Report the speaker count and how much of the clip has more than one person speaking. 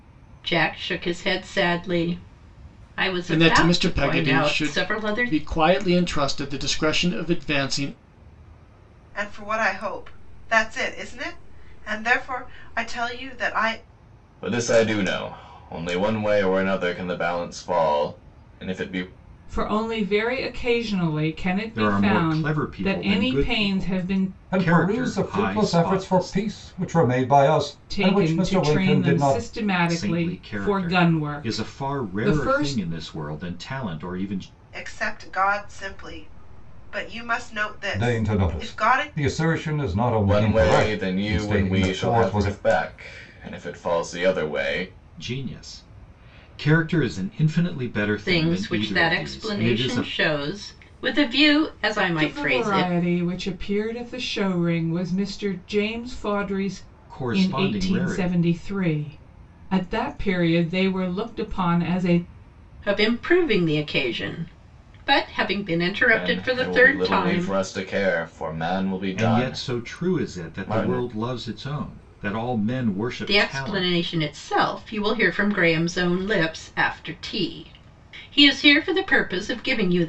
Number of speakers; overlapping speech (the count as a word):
seven, about 28%